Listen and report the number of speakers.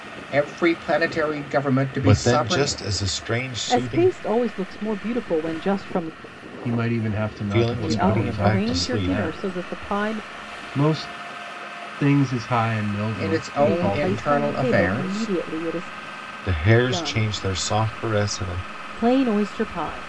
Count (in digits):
4